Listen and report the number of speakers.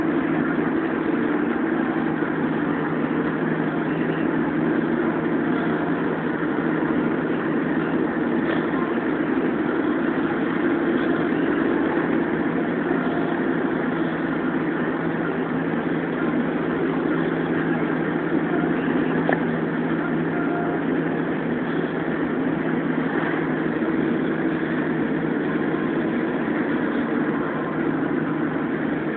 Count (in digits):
0